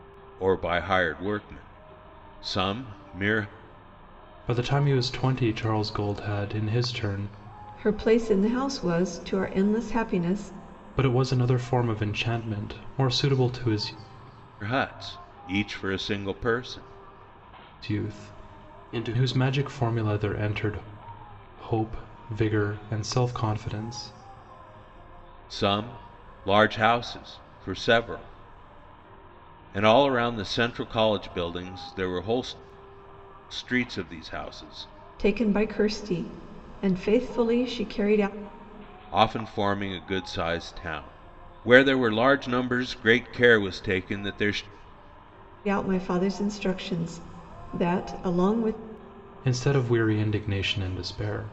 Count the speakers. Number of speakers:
three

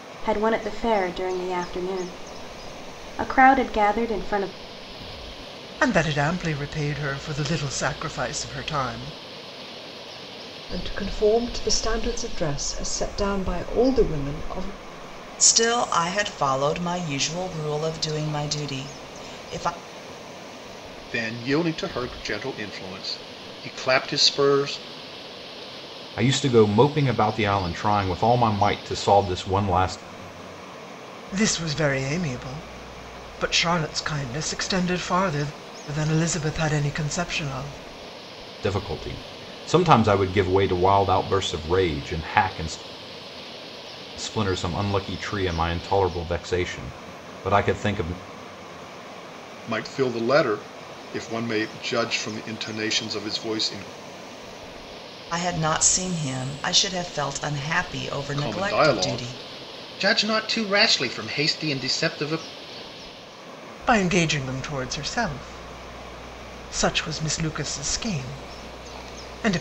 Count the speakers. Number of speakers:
six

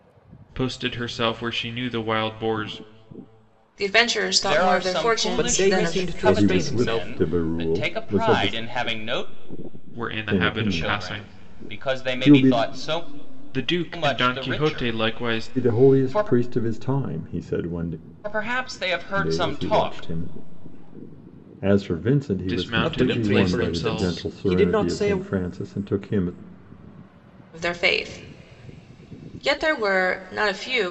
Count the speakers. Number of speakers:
five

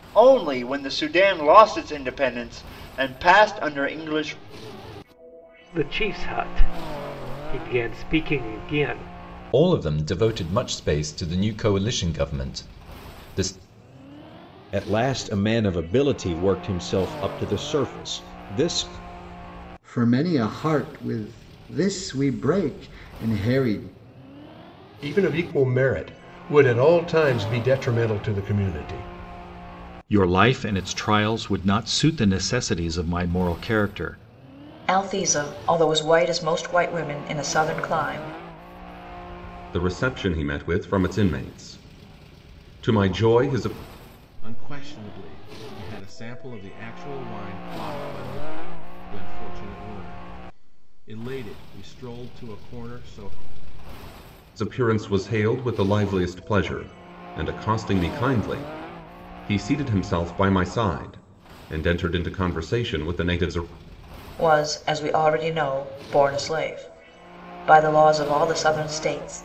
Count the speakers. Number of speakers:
ten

